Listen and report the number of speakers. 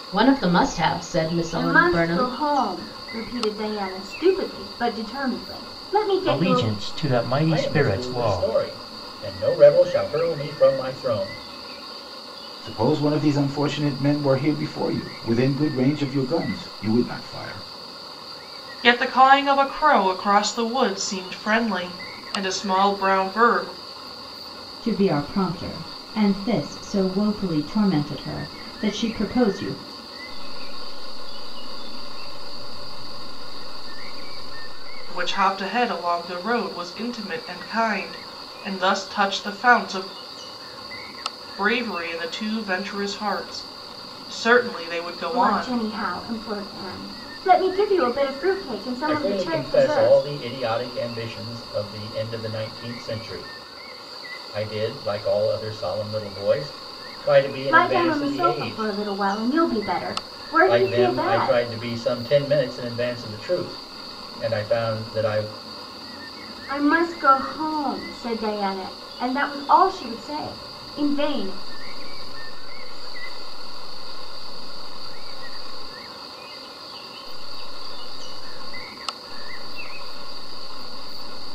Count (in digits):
8